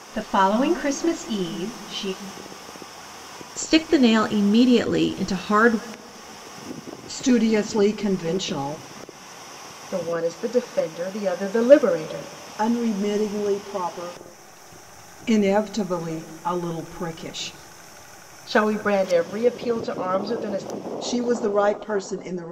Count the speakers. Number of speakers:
four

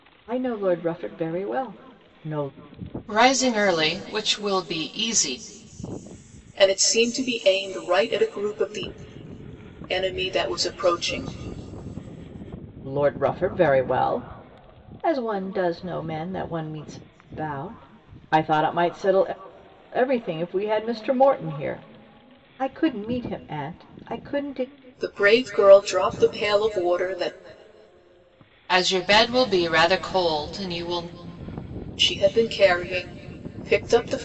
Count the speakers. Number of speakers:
three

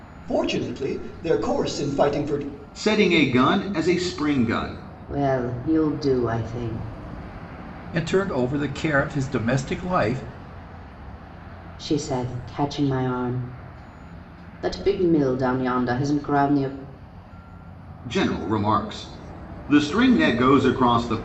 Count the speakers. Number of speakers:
four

